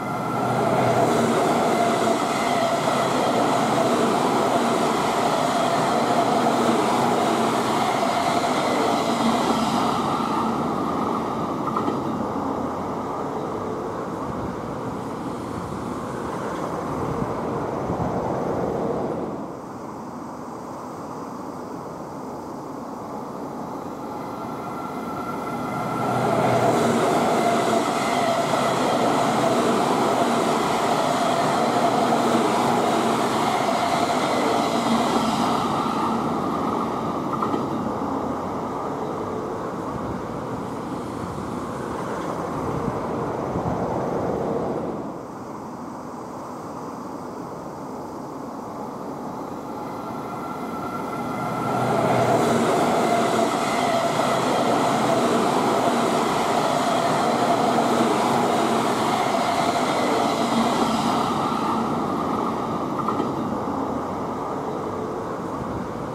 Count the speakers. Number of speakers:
0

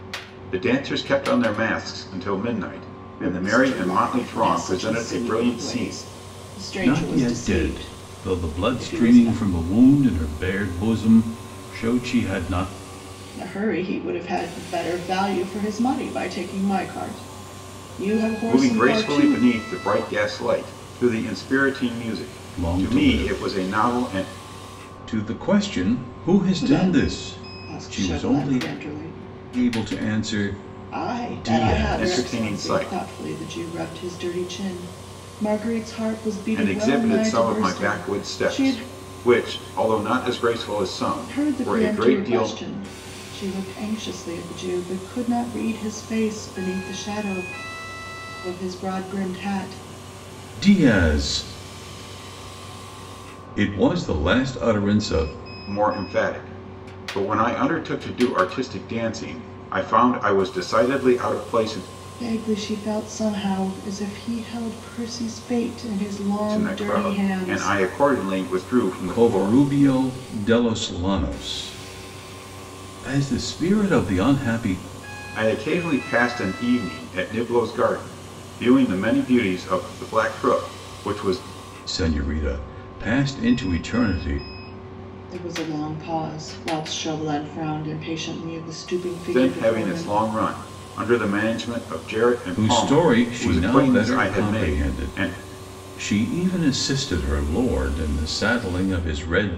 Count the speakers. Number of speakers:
3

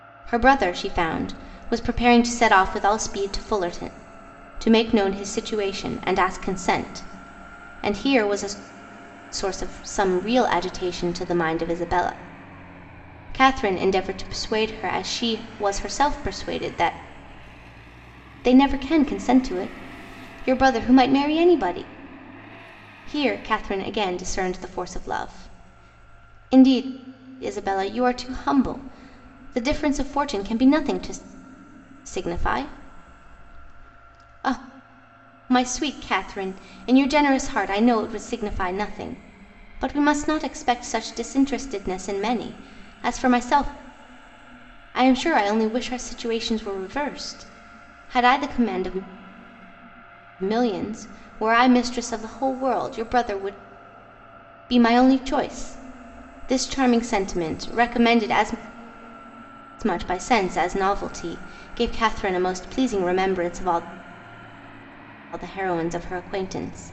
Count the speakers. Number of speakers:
1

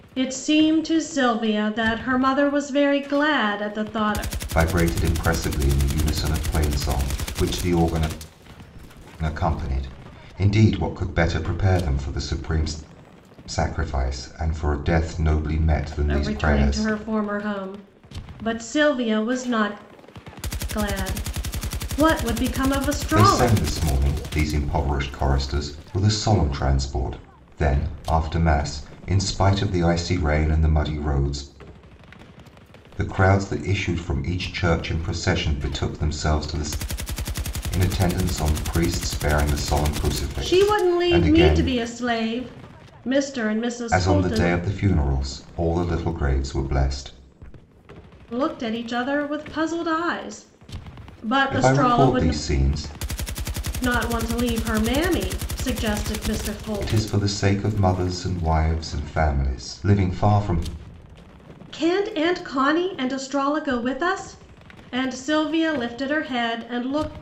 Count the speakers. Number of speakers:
2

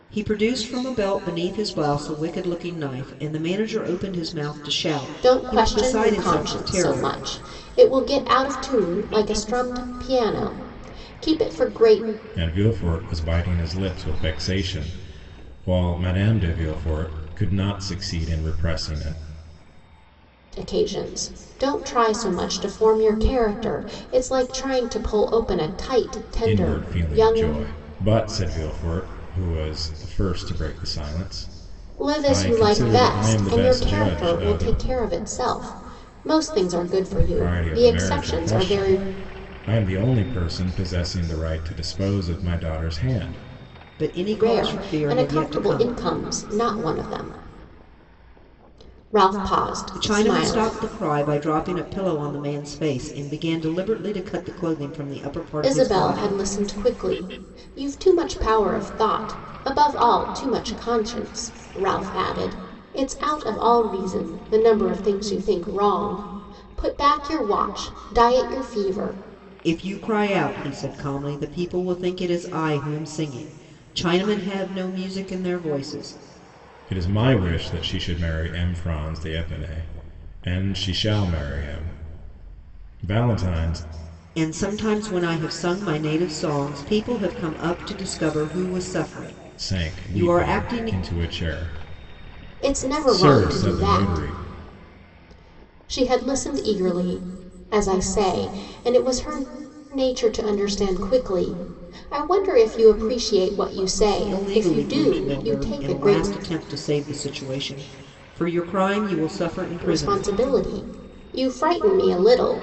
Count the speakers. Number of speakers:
3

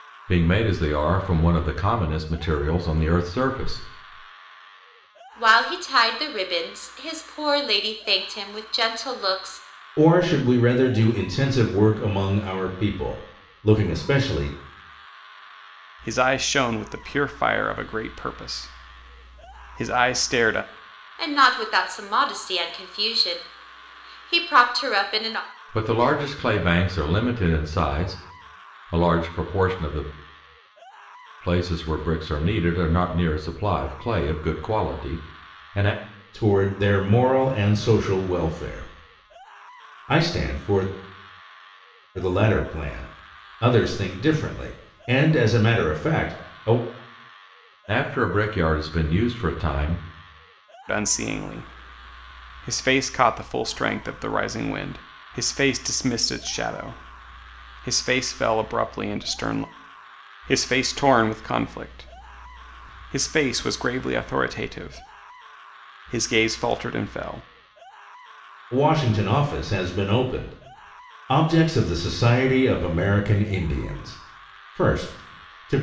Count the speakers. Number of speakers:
4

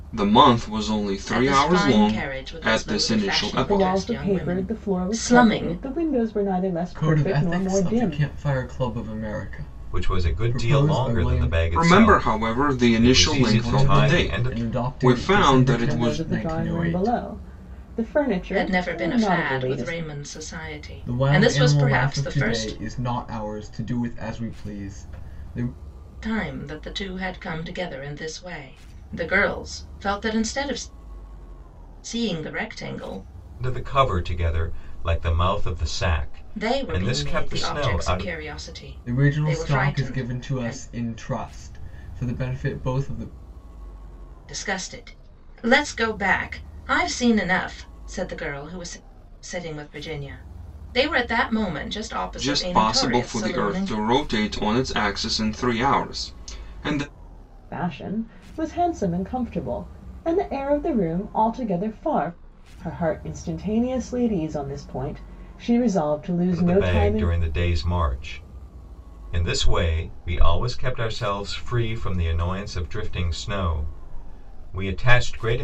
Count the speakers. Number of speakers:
5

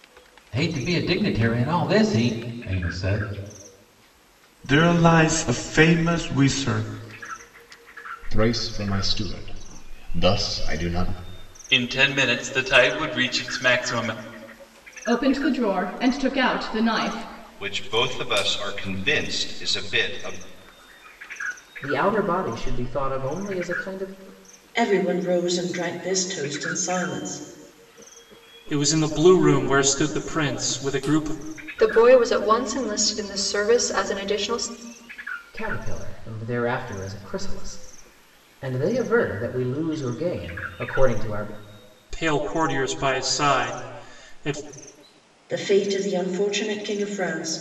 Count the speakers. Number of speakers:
10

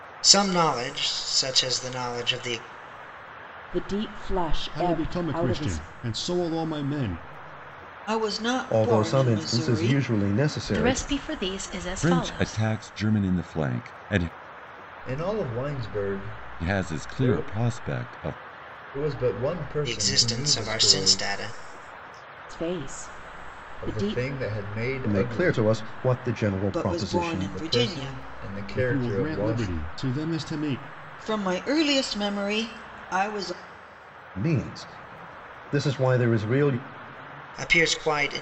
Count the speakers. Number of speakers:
8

